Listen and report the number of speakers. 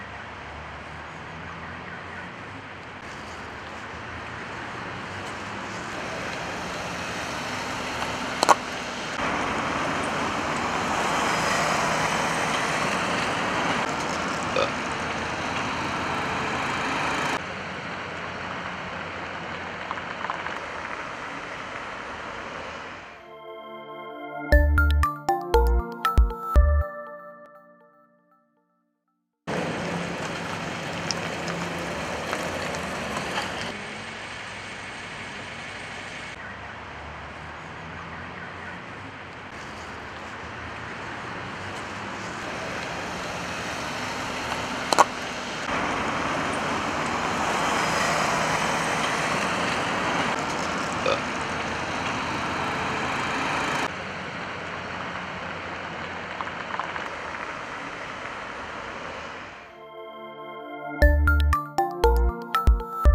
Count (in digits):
0